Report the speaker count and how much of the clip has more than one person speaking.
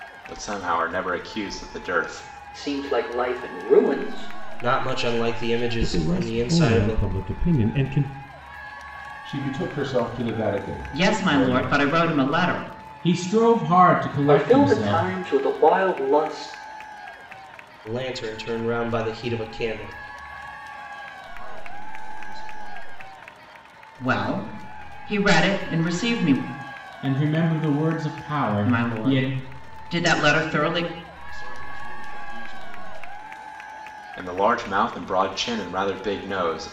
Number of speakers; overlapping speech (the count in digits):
8, about 14%